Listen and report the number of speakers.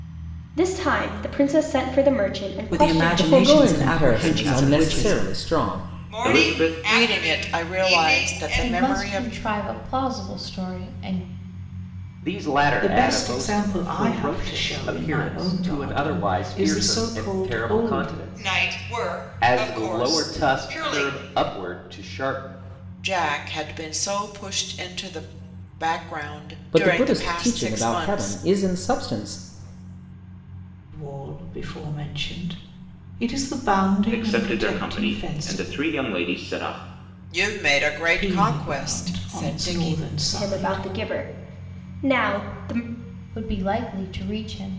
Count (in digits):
9